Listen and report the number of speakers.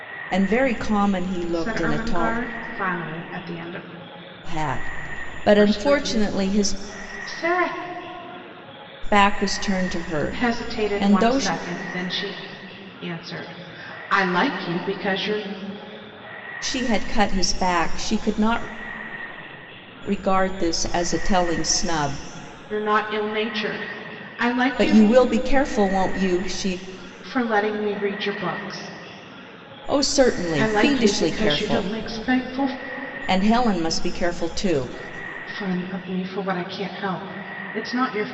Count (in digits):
2